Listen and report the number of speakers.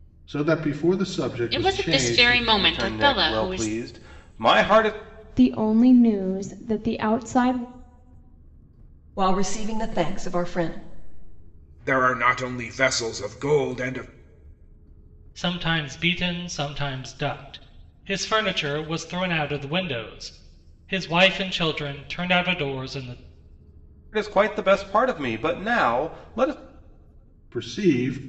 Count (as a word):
seven